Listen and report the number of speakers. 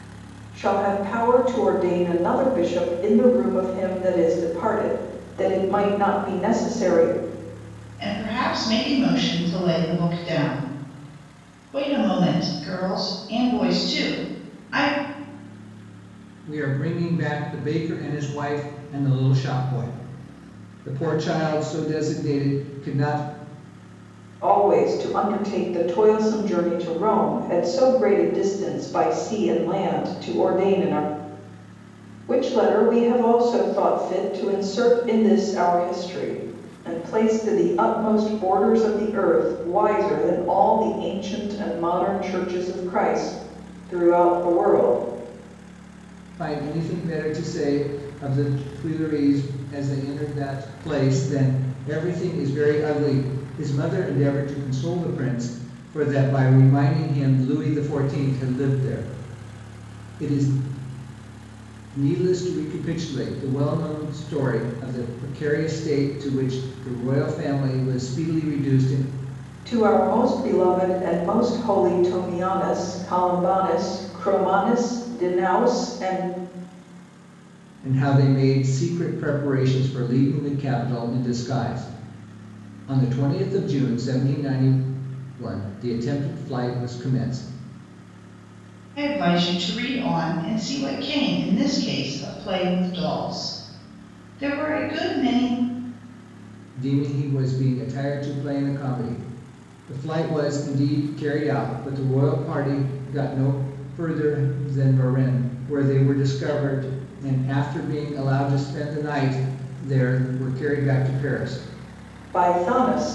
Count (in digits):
3